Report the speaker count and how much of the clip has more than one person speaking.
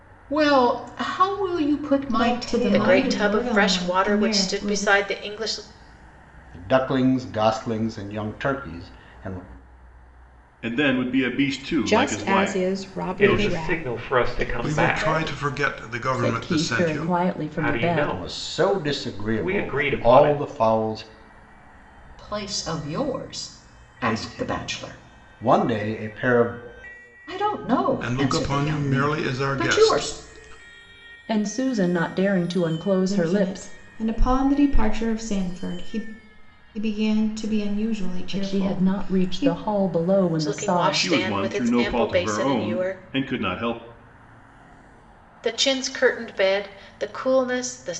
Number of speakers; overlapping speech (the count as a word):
ten, about 37%